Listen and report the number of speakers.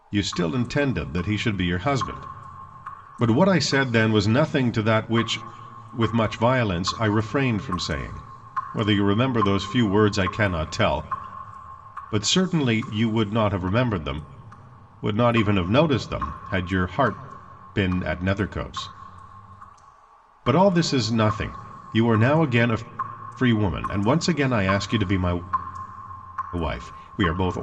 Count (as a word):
one